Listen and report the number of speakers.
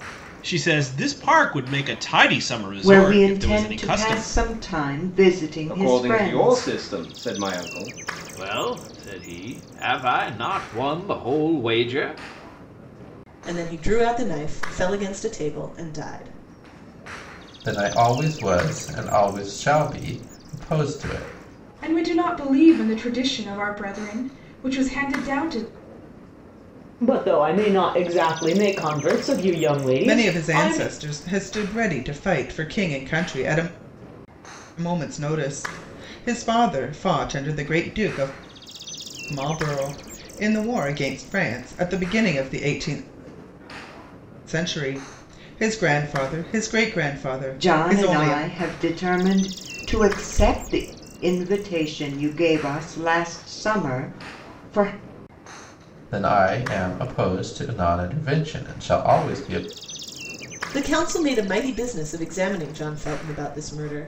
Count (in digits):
9